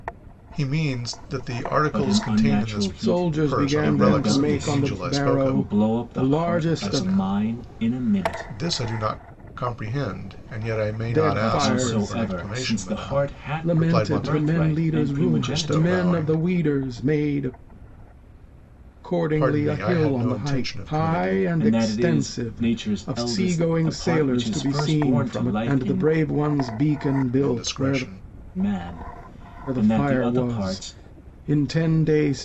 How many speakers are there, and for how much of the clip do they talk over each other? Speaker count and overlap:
3, about 63%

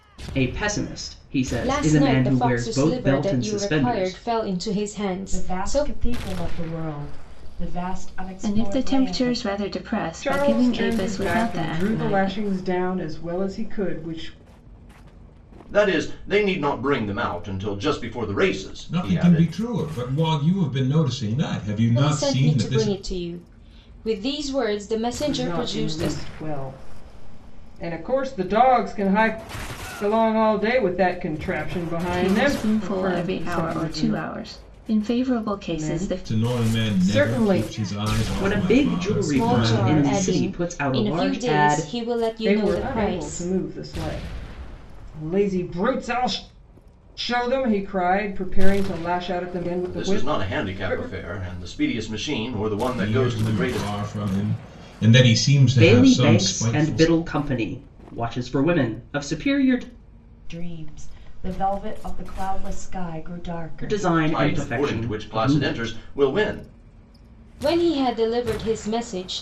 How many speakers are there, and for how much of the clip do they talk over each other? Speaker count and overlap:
7, about 34%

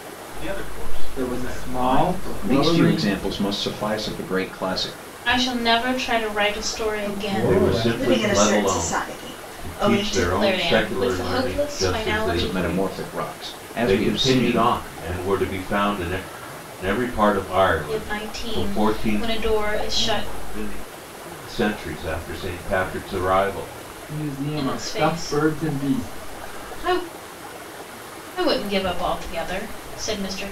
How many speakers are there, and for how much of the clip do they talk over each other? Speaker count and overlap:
7, about 44%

